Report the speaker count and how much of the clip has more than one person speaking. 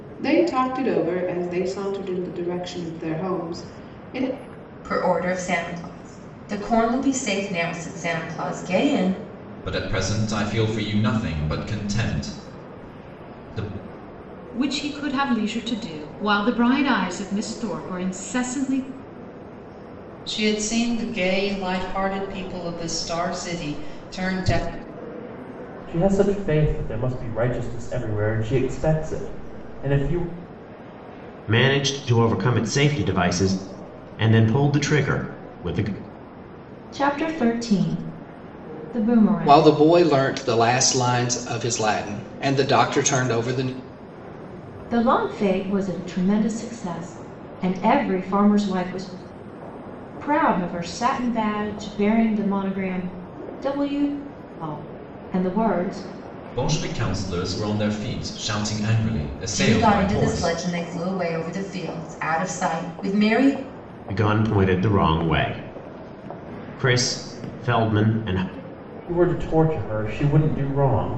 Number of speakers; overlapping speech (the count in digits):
9, about 2%